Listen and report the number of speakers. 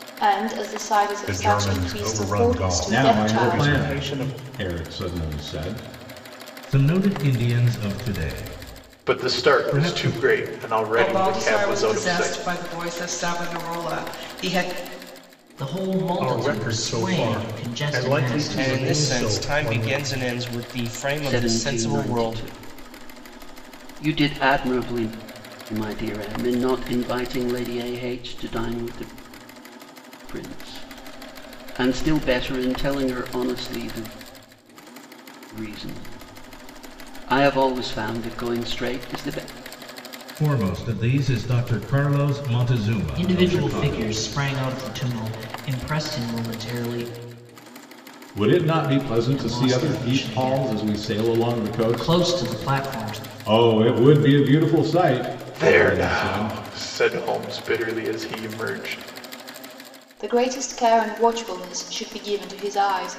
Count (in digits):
10